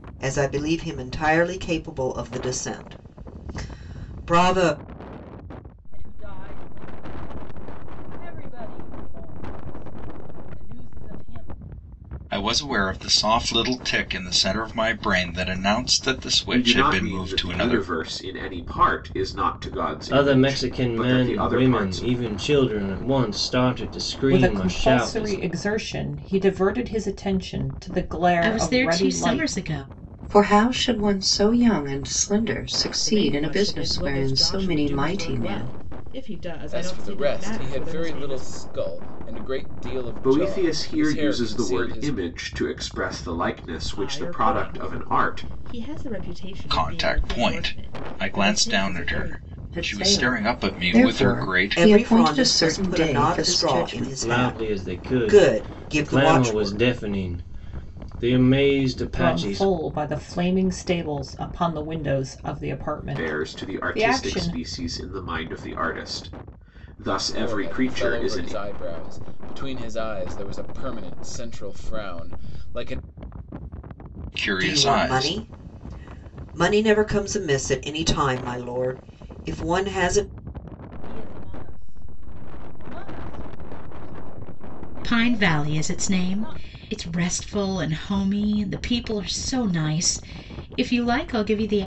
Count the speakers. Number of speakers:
10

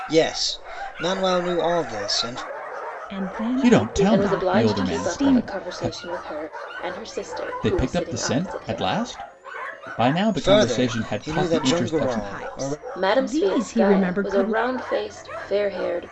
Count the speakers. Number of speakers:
4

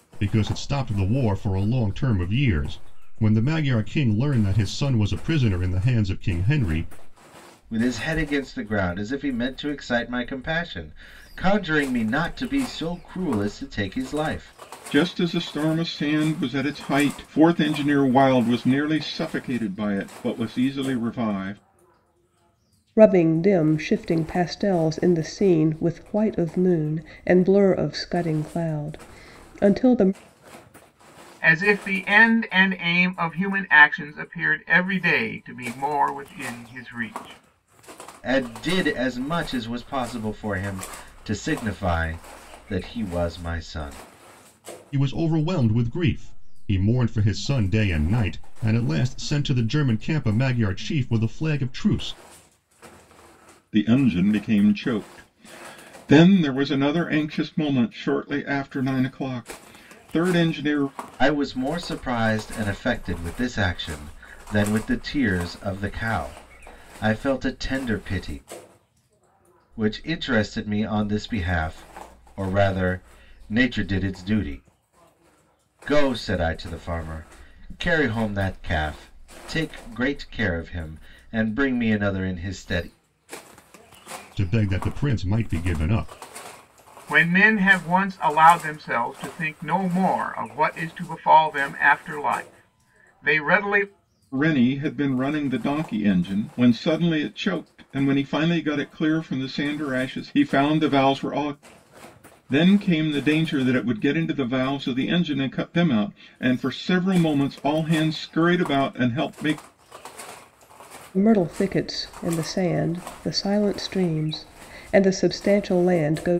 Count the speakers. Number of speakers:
5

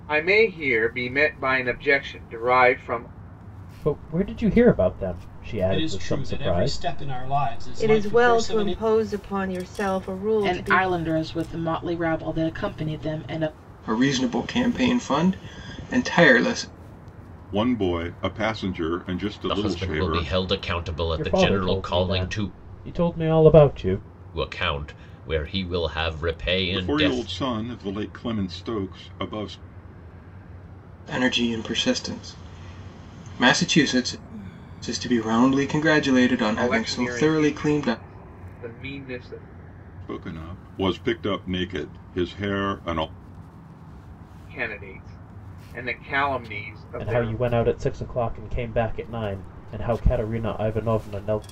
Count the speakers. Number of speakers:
8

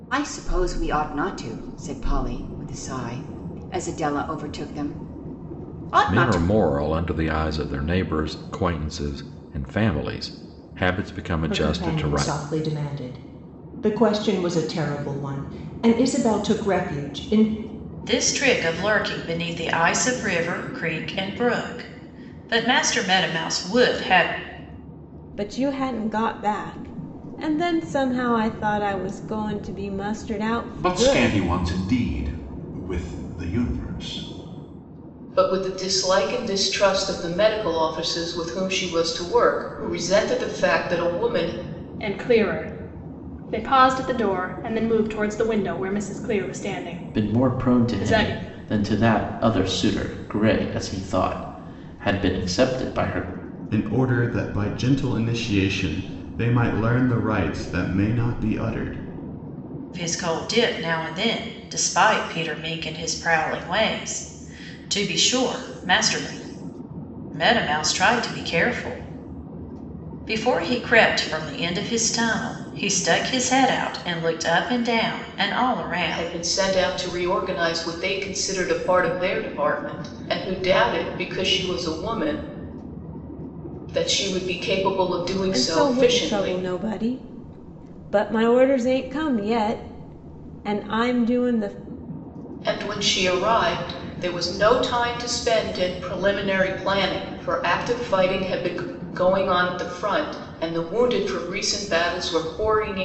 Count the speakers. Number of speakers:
10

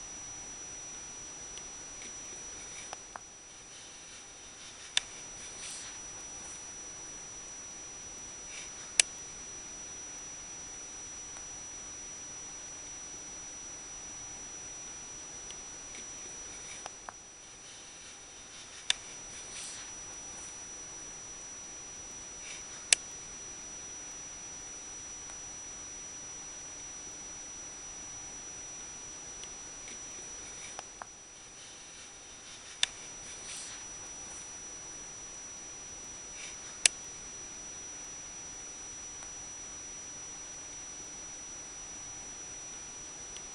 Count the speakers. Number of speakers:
0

